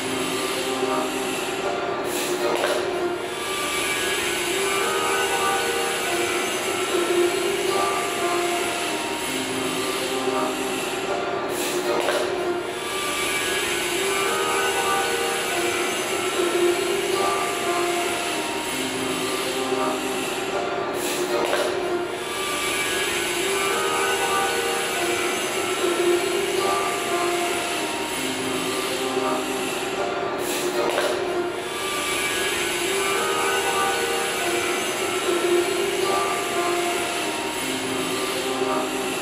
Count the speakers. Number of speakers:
0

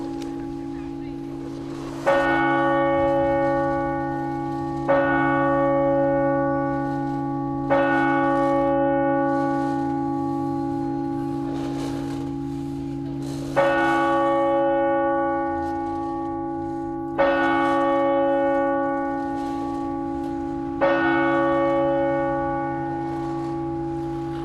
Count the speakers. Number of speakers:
0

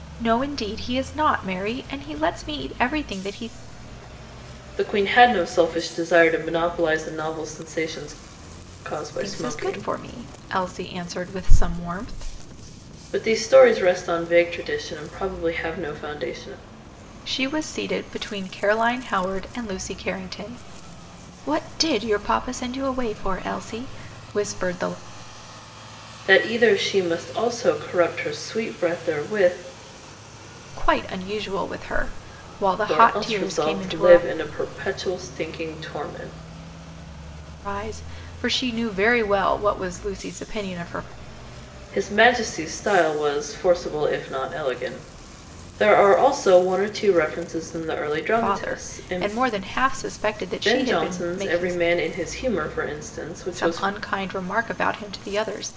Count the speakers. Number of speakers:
2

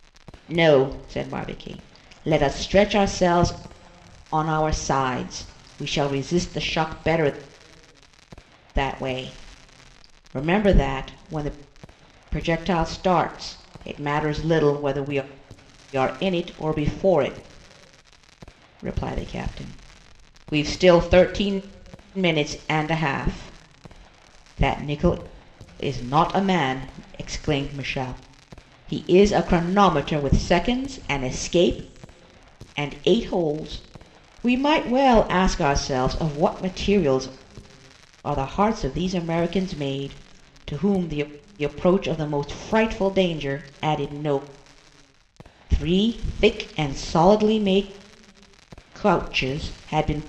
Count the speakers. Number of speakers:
1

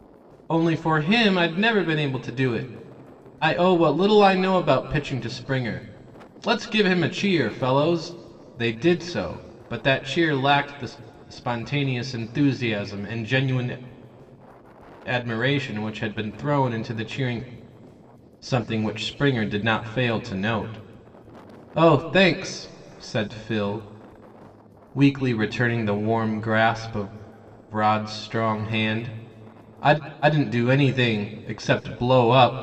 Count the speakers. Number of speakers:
1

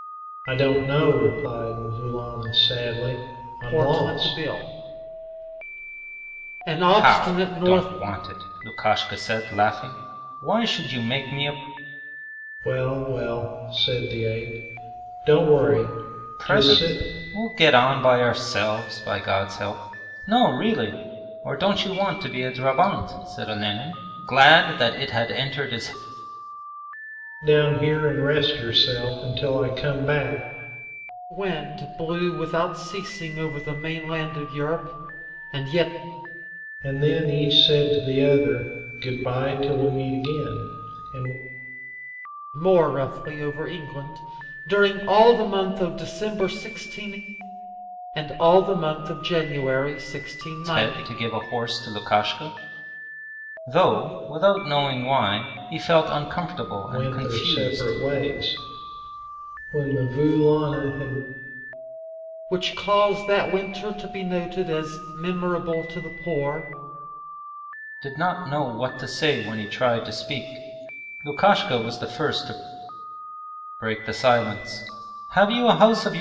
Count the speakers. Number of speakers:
3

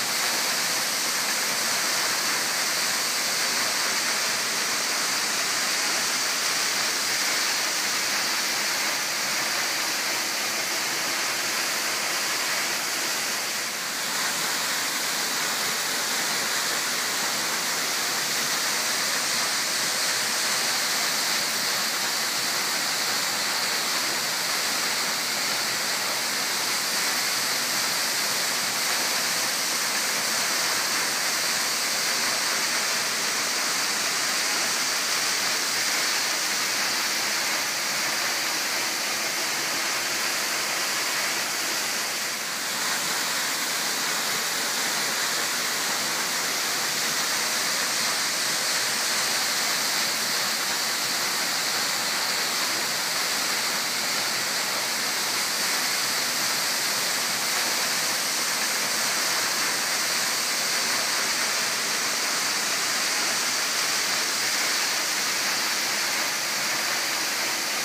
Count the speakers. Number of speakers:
0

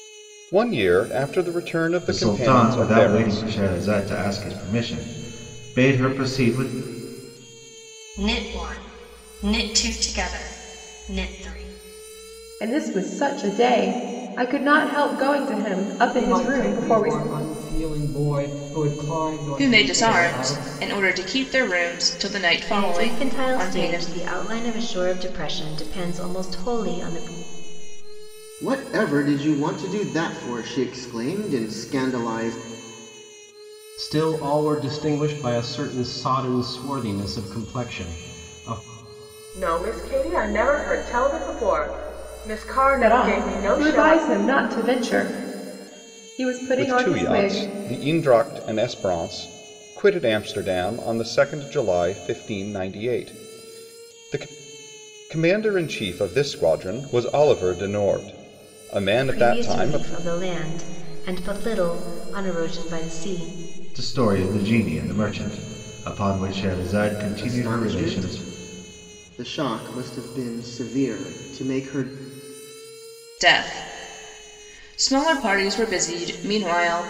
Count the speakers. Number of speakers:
10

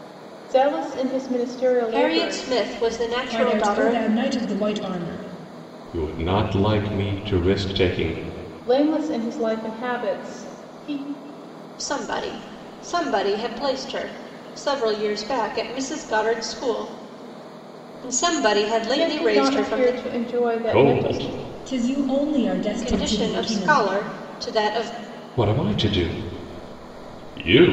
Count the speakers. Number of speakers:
4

